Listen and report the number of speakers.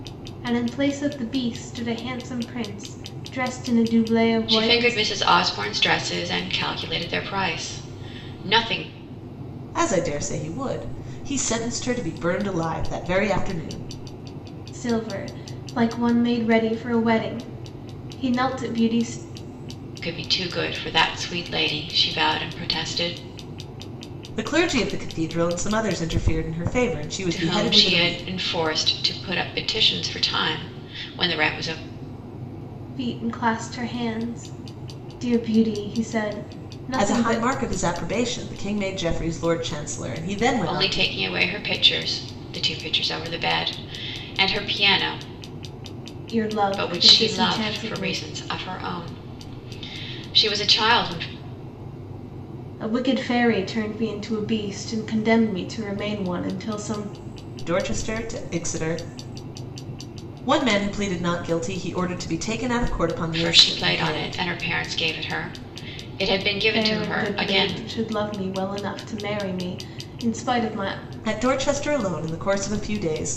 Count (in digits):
3